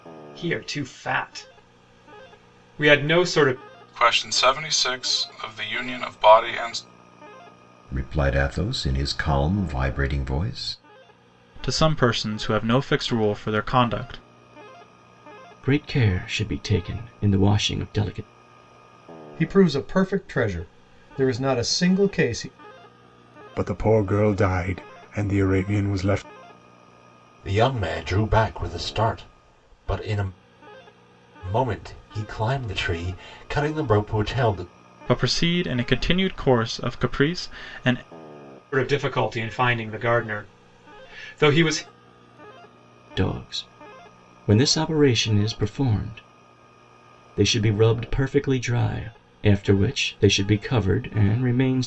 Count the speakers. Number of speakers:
8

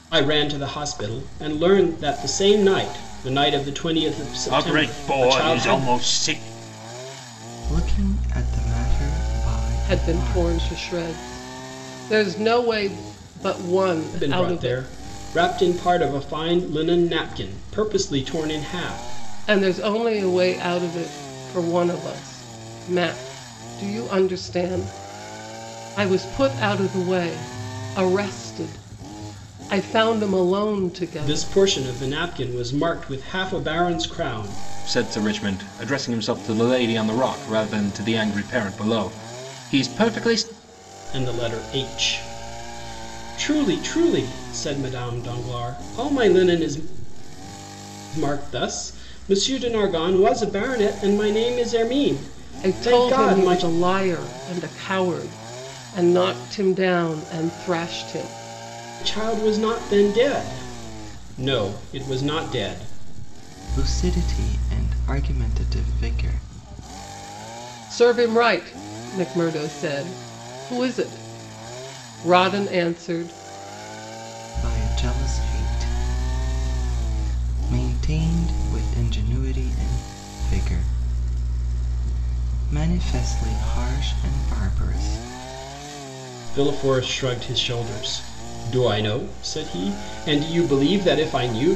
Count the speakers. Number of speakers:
4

